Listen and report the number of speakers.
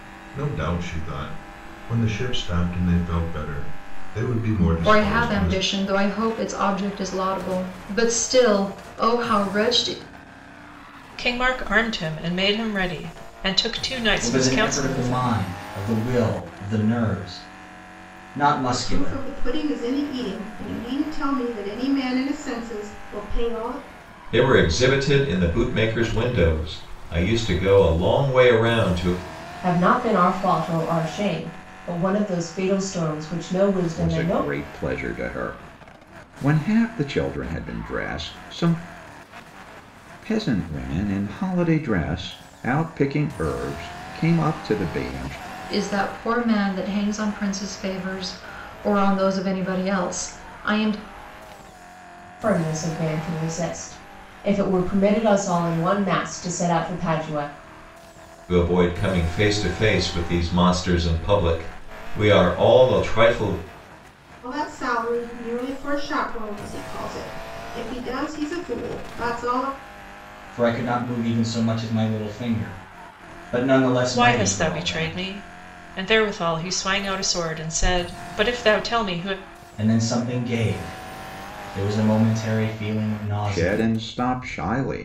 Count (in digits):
8